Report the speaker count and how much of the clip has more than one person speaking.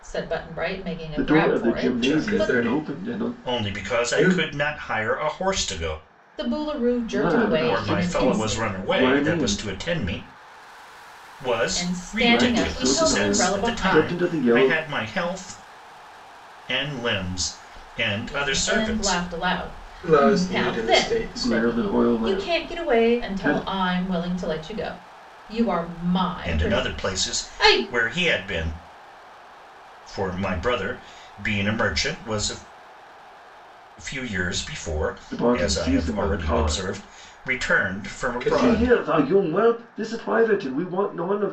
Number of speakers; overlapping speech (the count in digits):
4, about 41%